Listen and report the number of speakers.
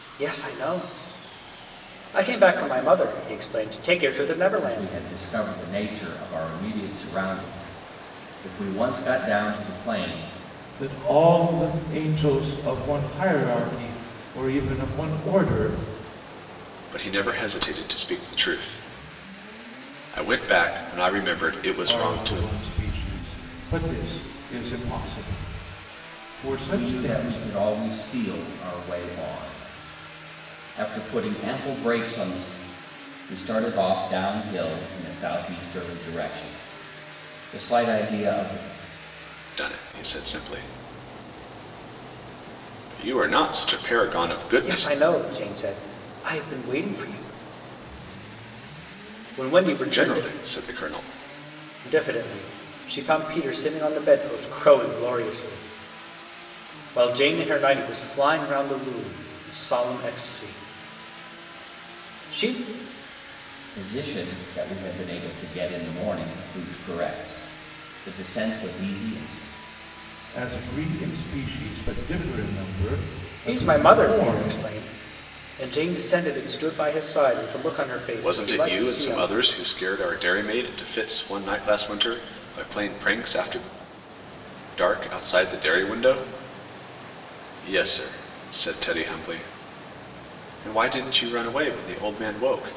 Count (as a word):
four